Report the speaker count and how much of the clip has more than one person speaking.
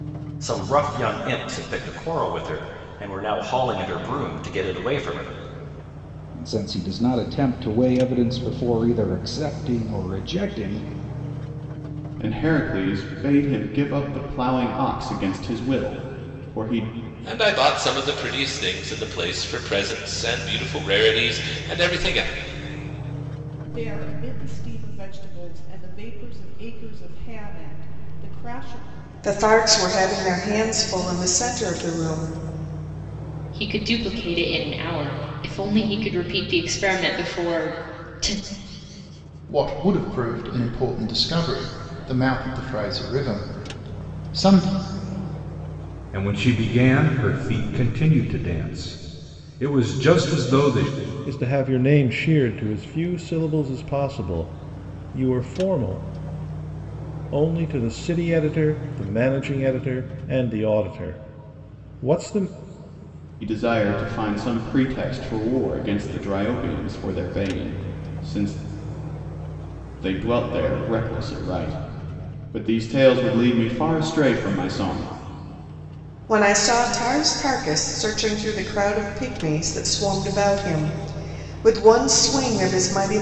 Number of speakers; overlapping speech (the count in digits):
10, no overlap